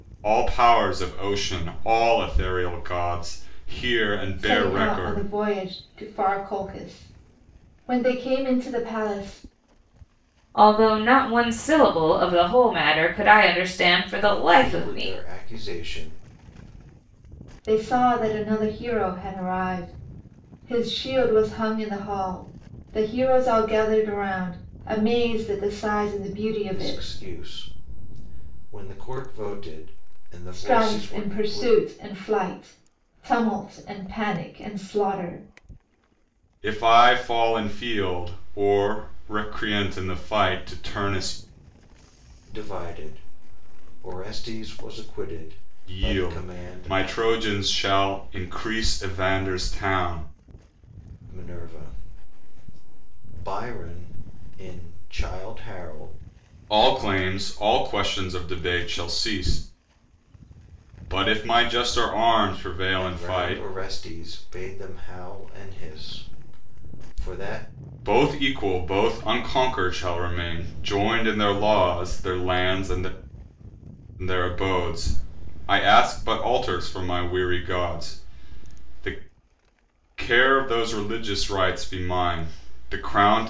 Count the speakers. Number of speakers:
4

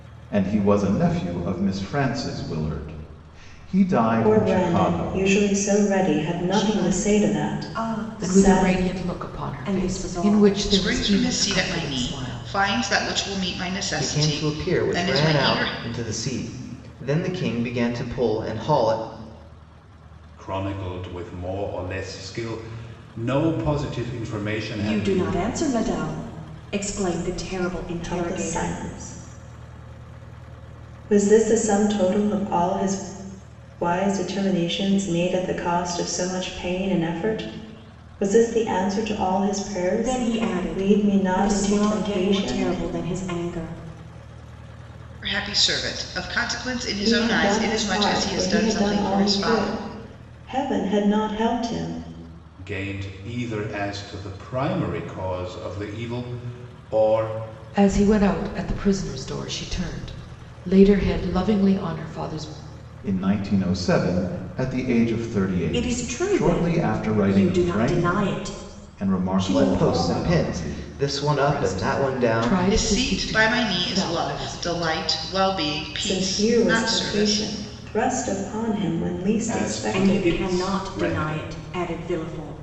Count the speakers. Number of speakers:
7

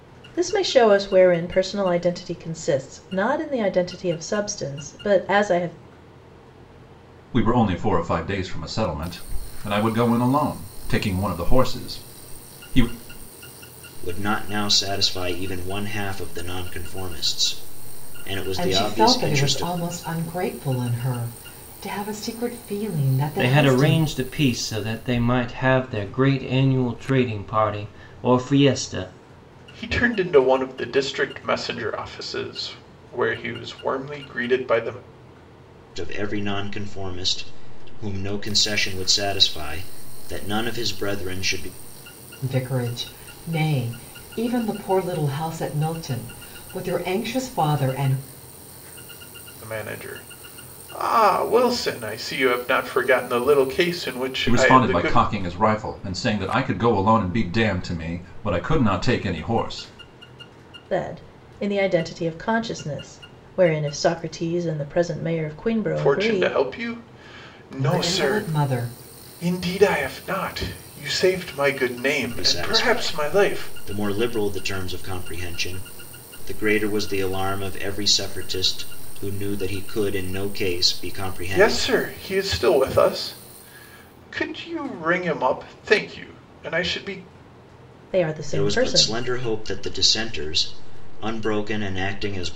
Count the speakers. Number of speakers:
6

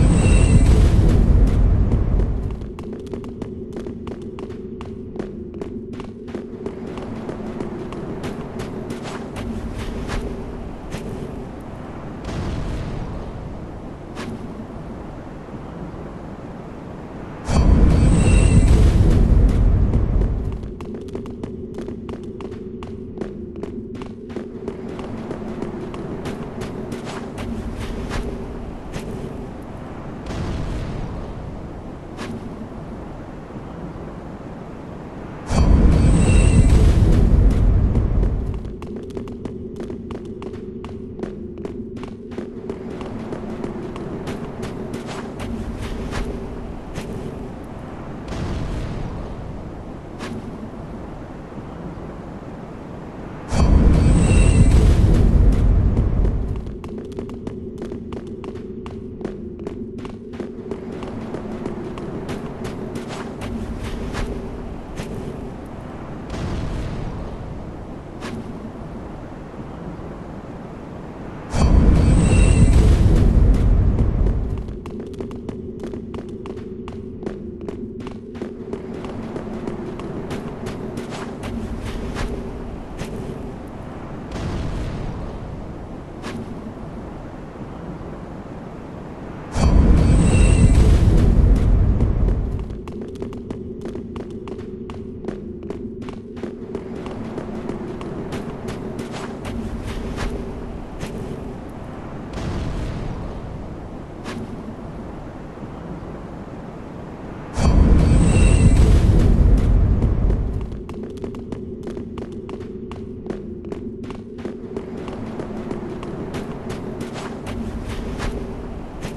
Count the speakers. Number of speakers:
0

